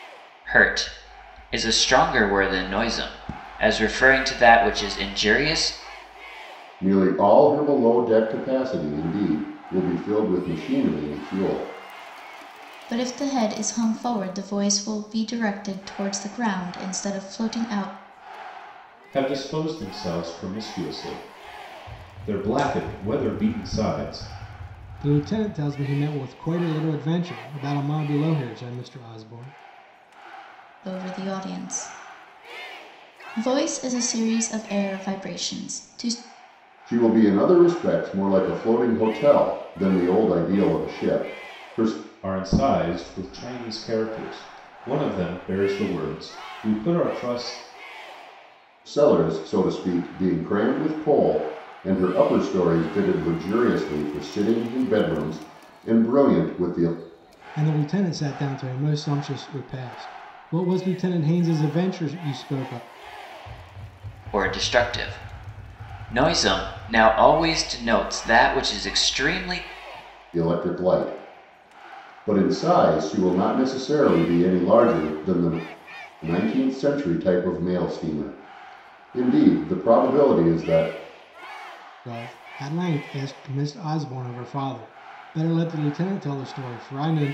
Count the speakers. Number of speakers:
5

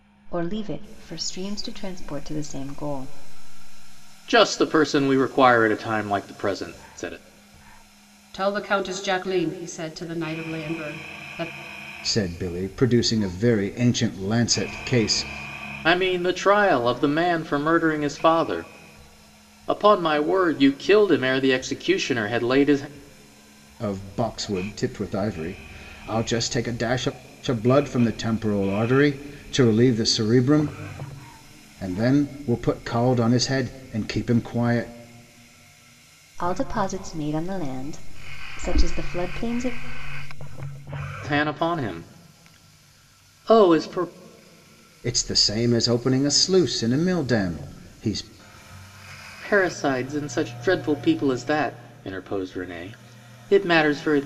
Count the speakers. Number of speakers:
4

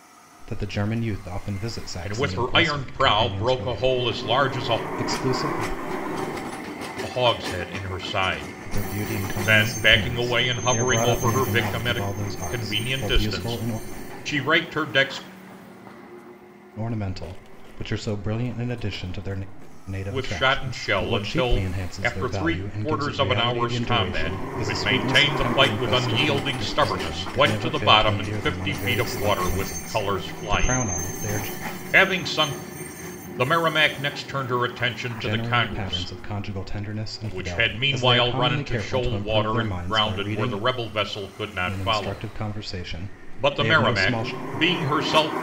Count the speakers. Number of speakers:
2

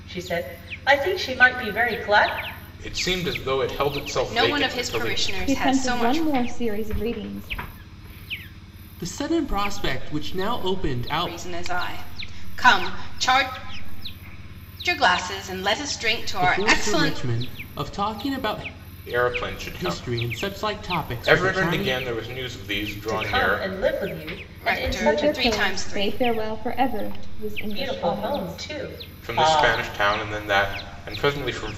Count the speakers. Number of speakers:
6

